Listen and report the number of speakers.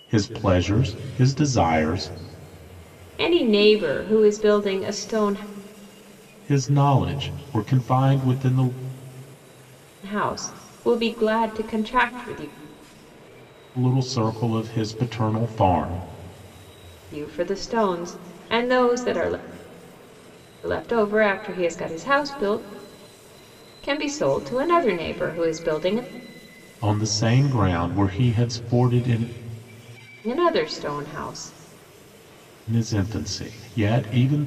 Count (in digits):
2